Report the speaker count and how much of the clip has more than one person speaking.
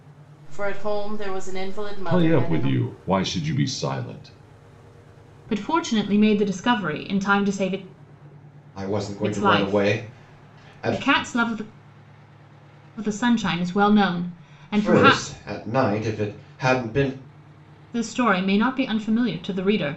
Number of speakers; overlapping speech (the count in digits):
4, about 16%